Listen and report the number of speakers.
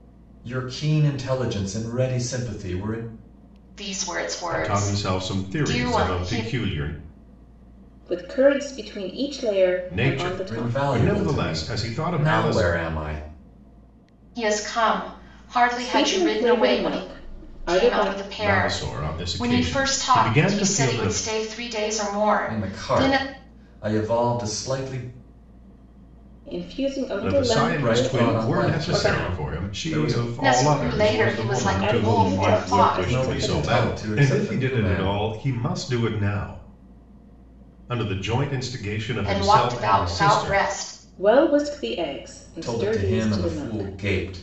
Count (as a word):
four